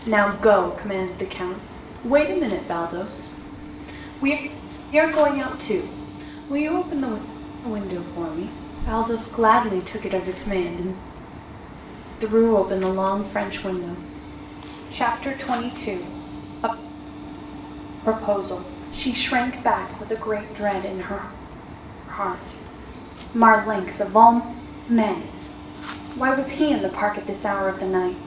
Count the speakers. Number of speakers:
1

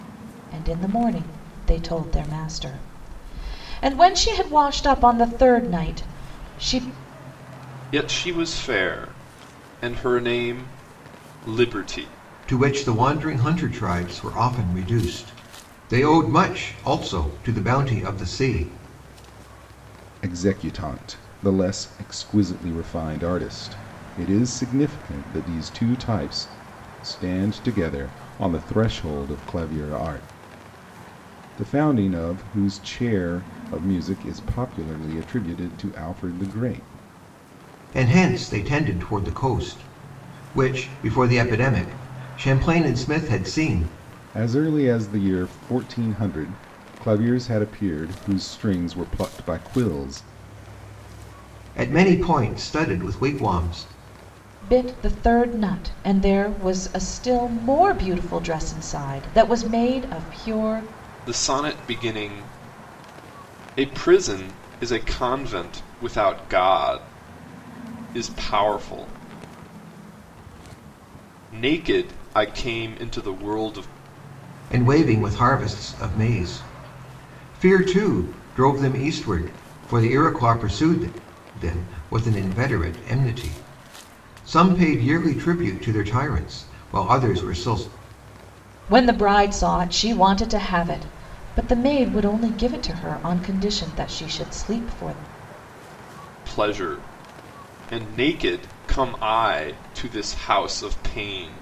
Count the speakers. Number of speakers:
4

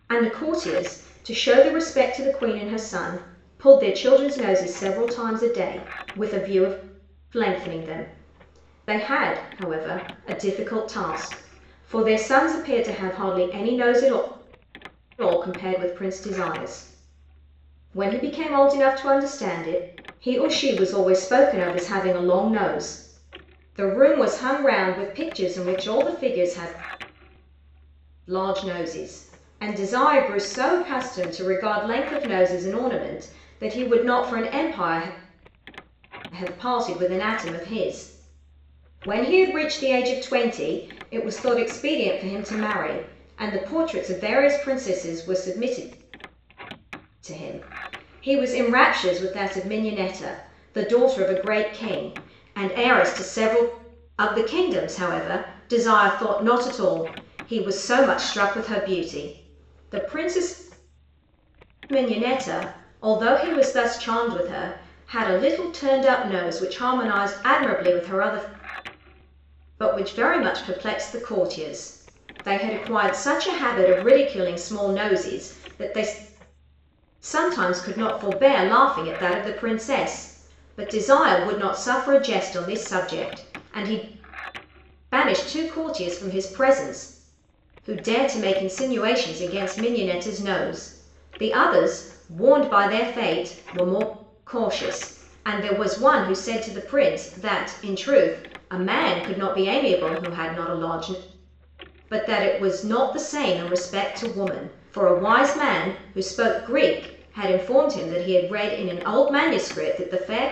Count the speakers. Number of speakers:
1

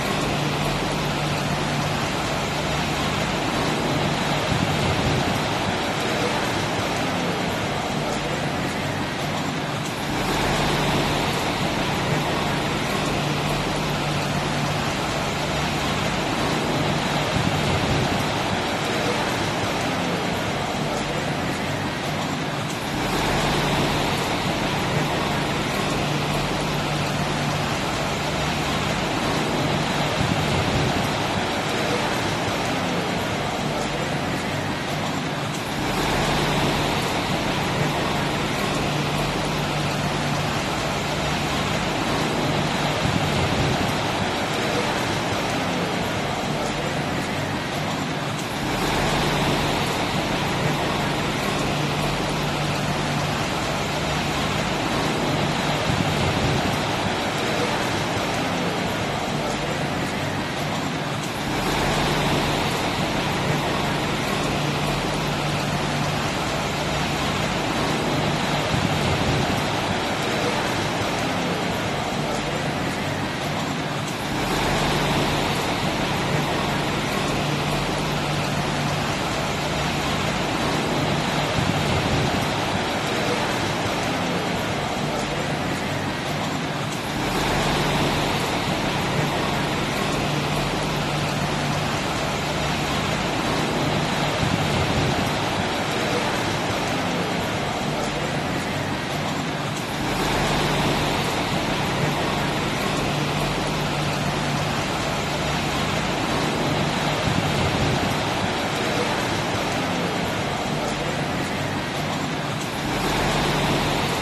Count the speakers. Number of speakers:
0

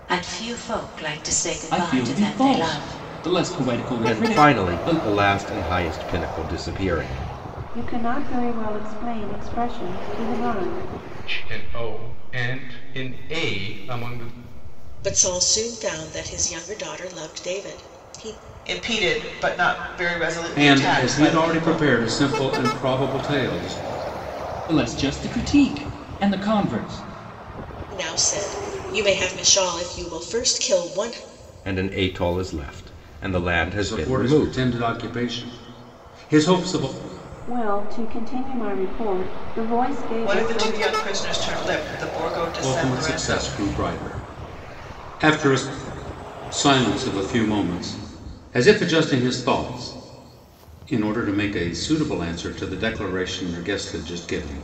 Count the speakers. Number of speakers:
8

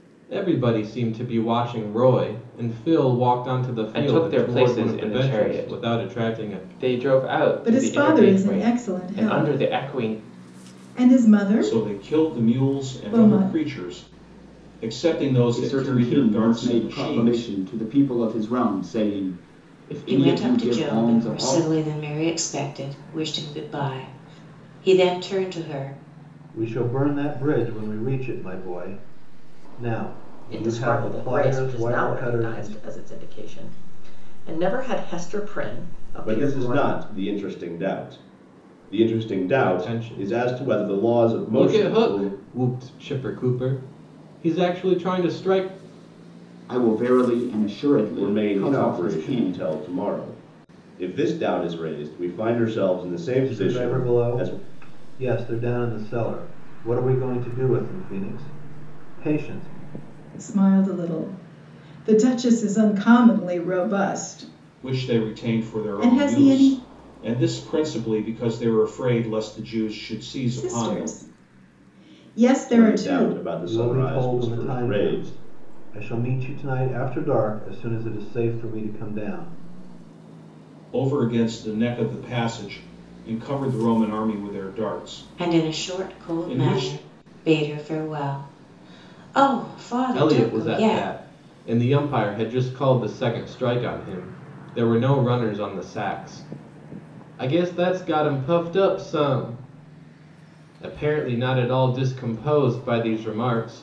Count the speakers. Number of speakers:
9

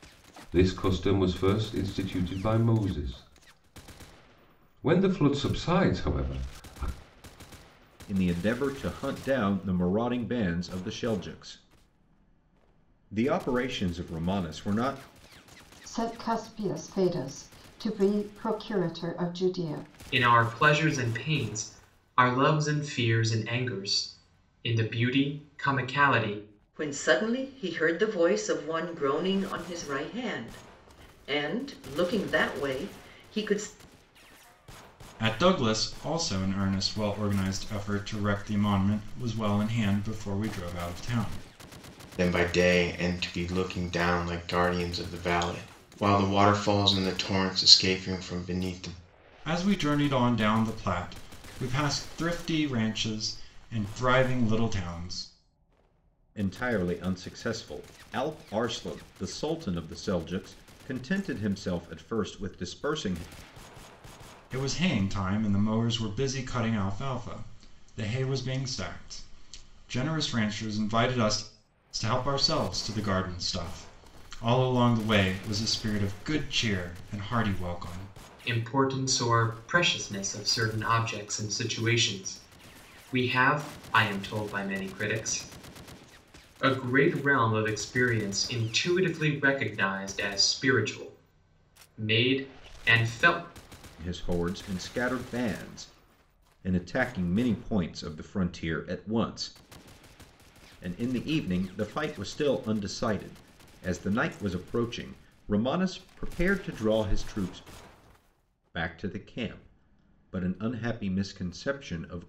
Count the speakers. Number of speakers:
7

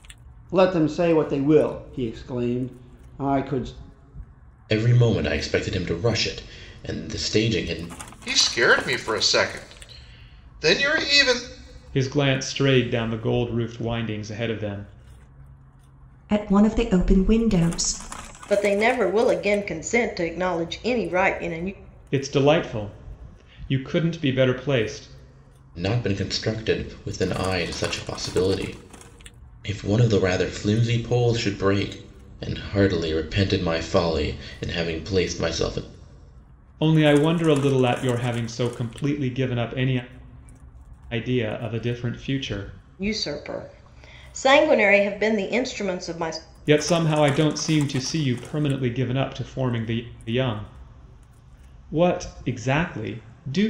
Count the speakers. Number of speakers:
6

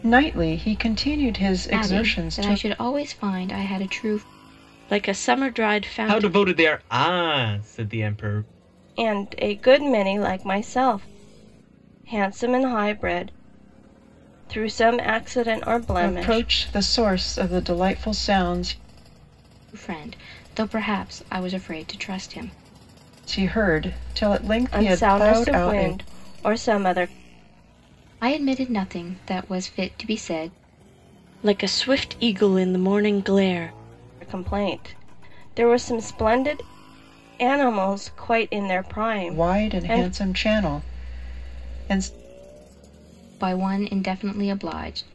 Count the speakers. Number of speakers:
5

